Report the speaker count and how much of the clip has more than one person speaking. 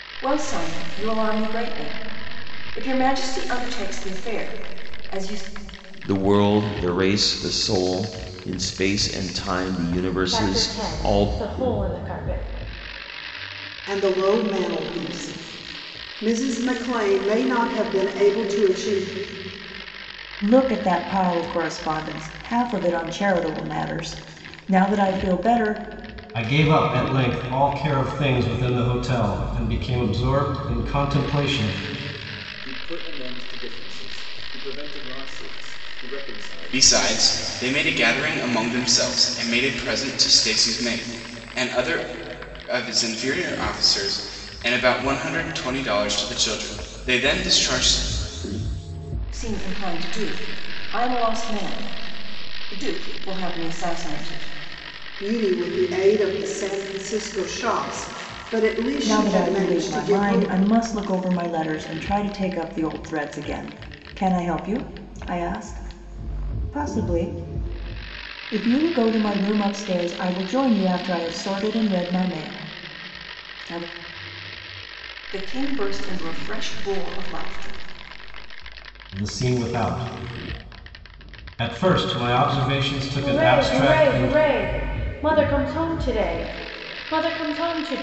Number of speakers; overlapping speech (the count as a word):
eight, about 5%